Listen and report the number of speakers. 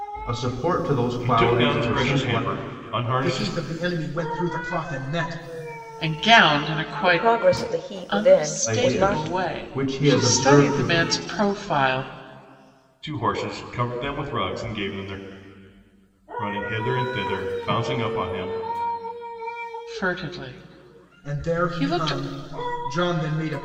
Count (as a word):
five